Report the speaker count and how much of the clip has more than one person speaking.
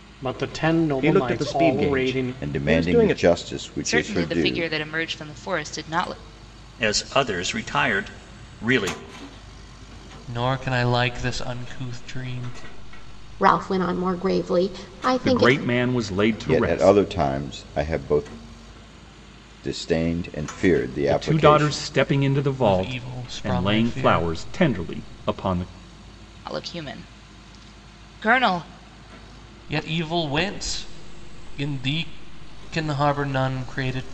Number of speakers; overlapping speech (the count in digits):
8, about 19%